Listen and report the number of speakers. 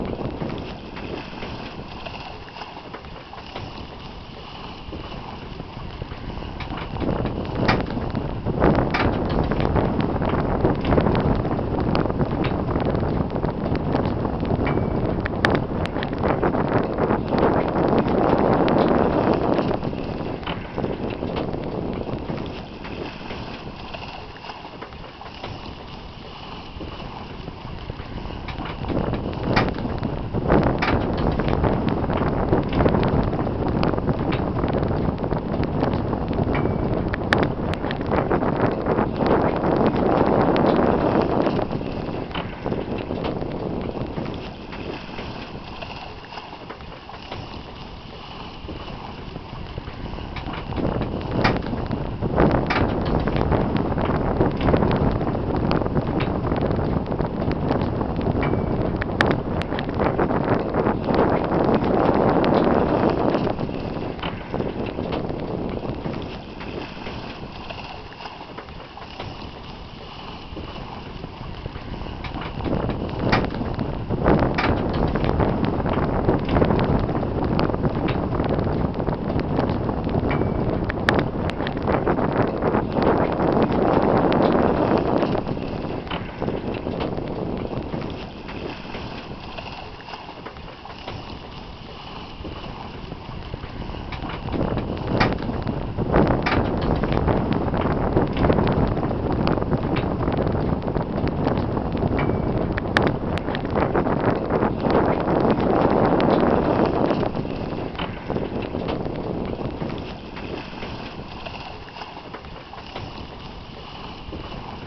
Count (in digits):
0